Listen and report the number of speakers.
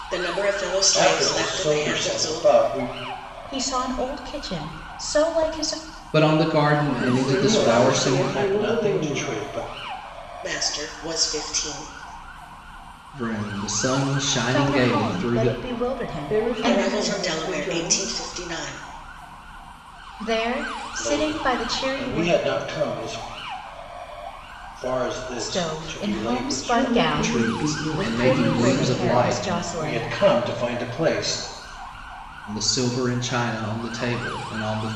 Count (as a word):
five